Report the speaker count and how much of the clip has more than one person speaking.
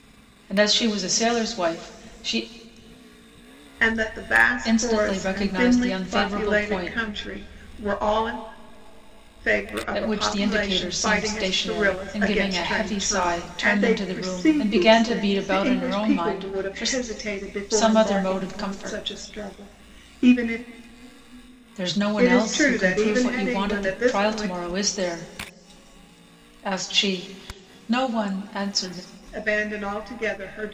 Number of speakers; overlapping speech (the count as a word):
two, about 43%